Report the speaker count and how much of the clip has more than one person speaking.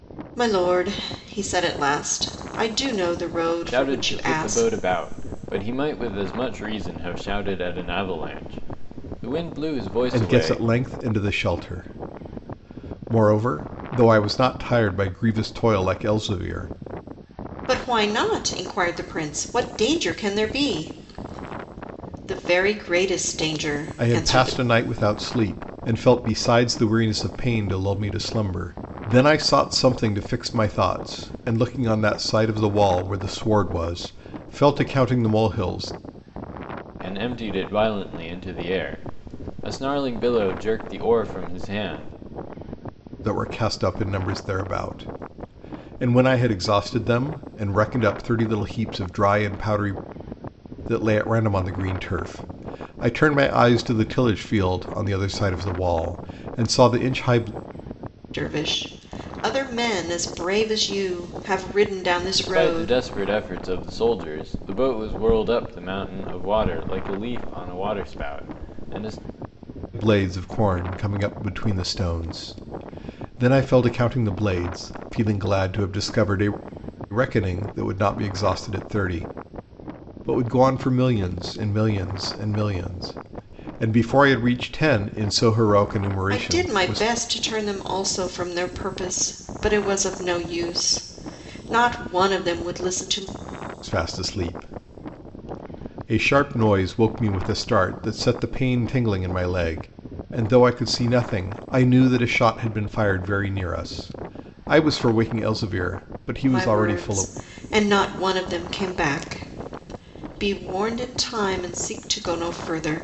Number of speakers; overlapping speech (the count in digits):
3, about 4%